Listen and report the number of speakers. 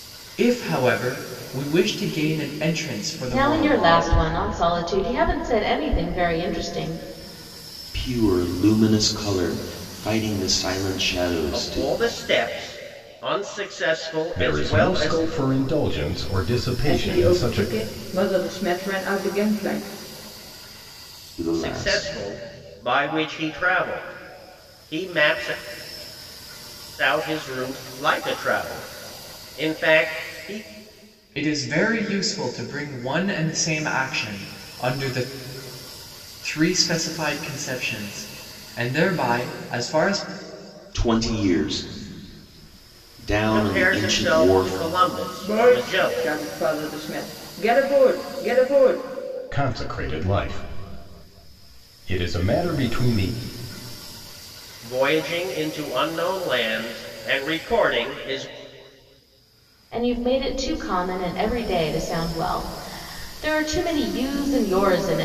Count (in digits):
6